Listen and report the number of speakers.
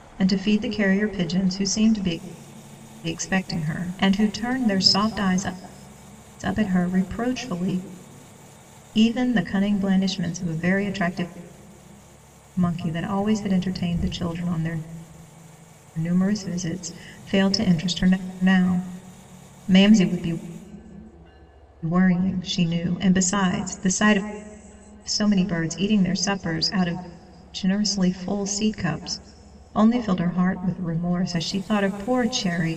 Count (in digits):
1